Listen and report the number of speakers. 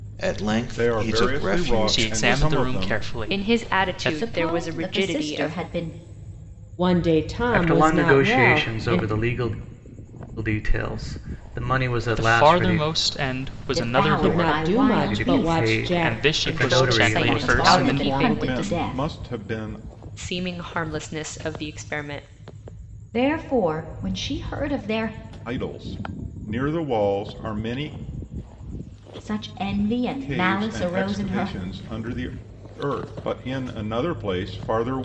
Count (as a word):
seven